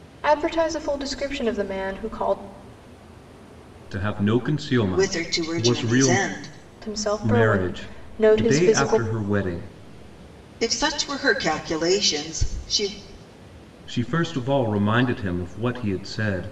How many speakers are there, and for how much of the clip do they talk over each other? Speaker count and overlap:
3, about 19%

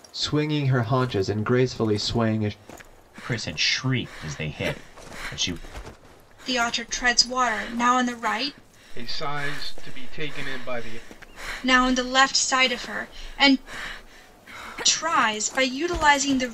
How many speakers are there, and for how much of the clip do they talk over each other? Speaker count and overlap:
4, no overlap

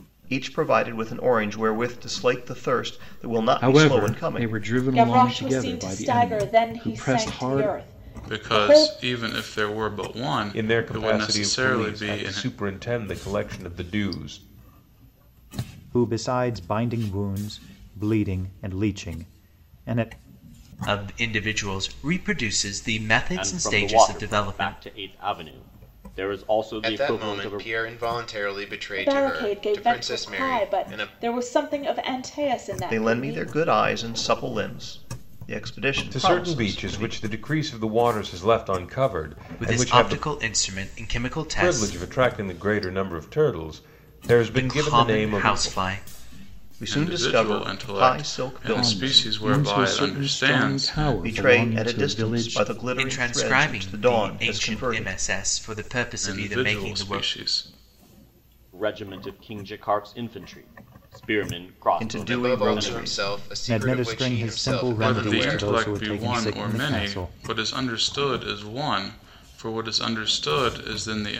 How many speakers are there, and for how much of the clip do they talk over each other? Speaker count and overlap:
9, about 42%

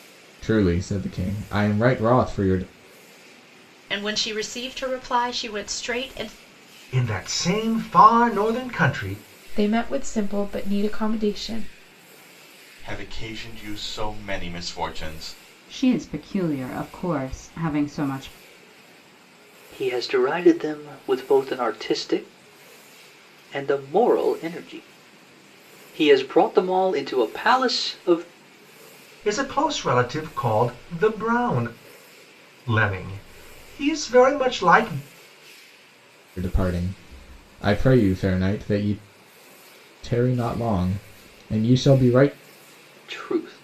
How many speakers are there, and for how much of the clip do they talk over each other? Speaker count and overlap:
7, no overlap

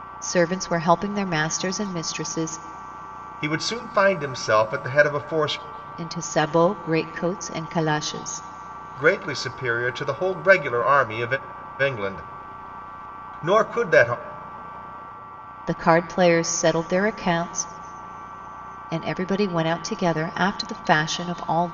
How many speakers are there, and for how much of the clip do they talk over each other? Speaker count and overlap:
2, no overlap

